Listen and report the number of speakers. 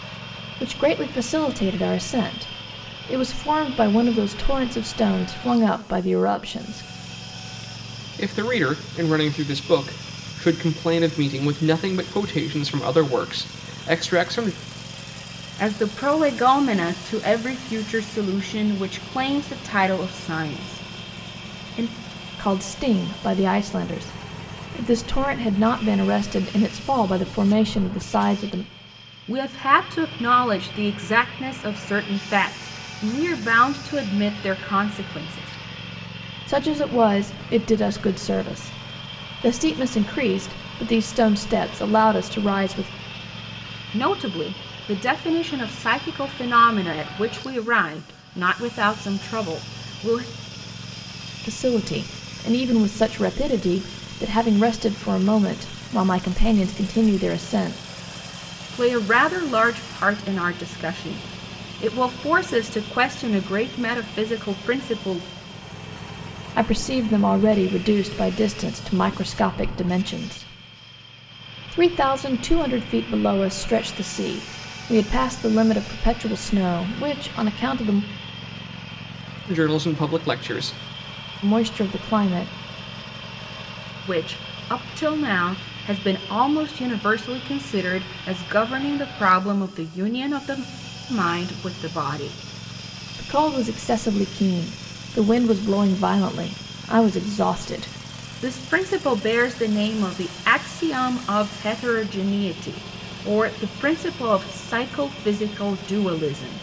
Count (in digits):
3